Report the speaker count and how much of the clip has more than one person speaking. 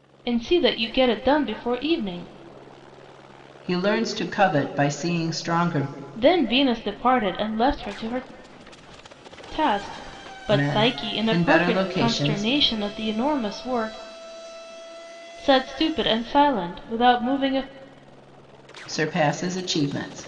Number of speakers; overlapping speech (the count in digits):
2, about 10%